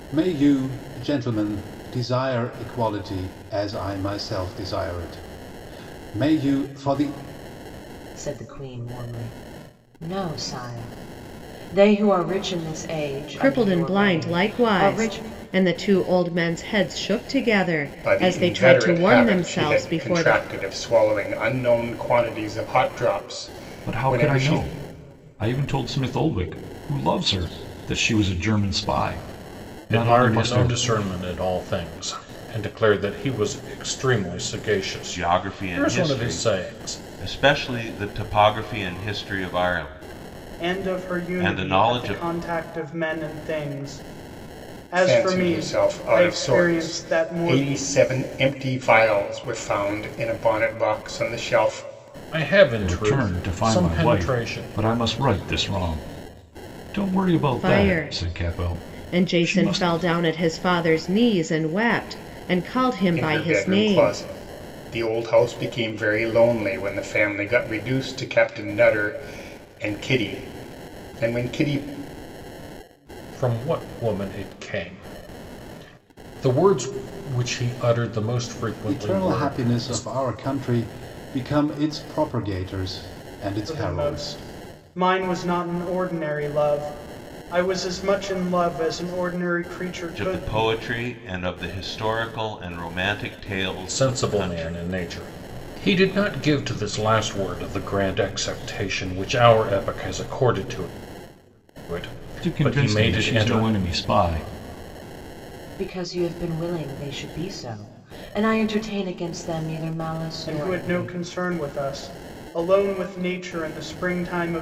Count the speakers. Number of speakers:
eight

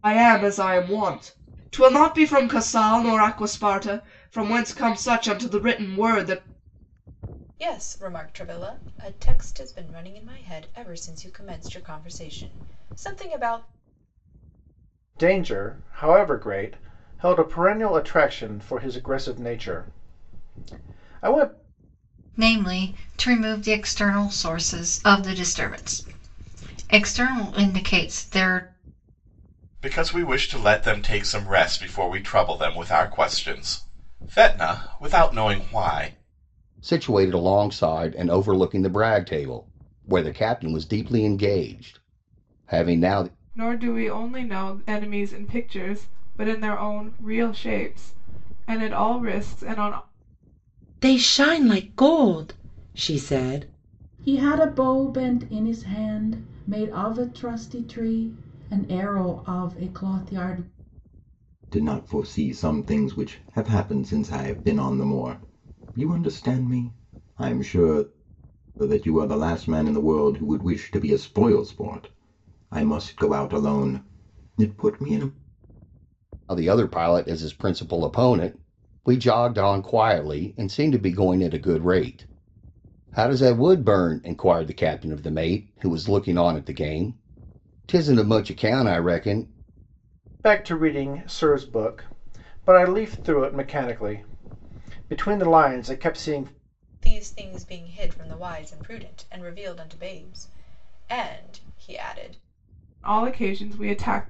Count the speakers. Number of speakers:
ten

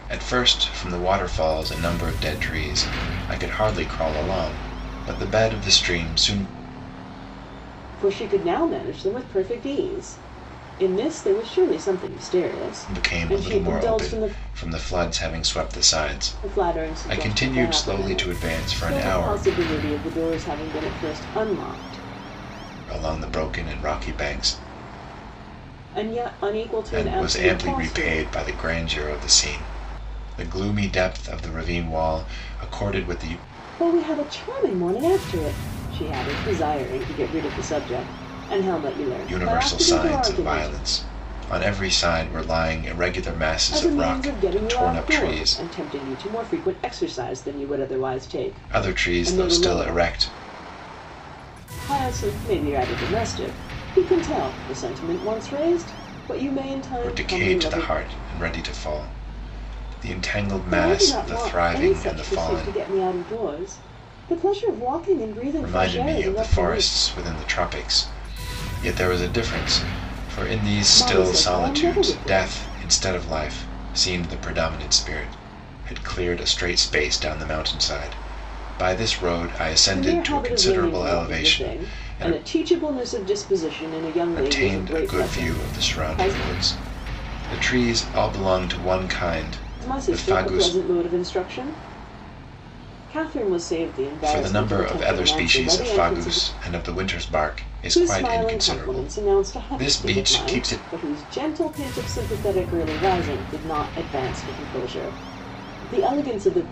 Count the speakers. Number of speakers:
two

